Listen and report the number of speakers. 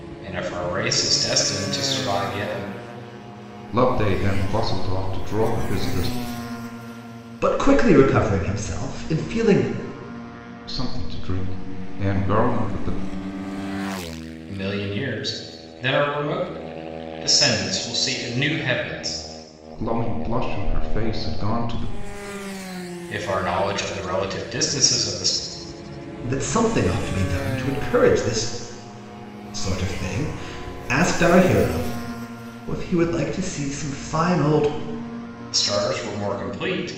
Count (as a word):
three